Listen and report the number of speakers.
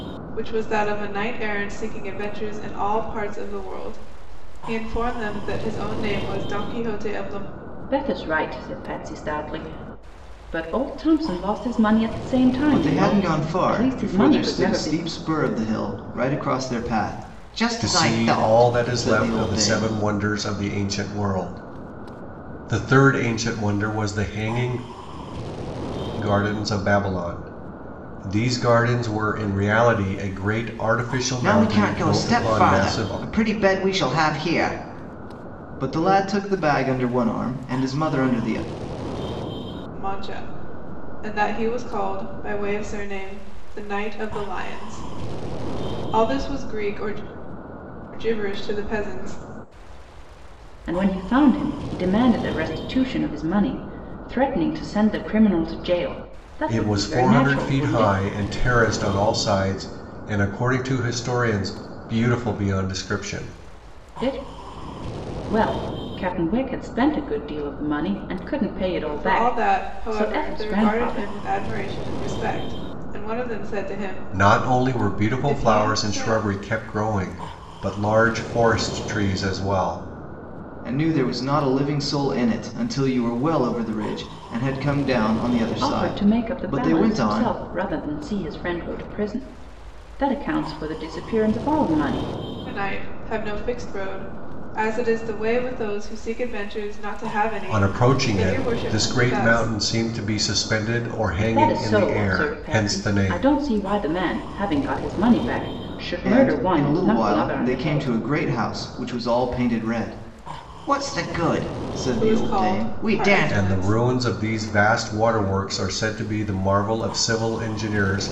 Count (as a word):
four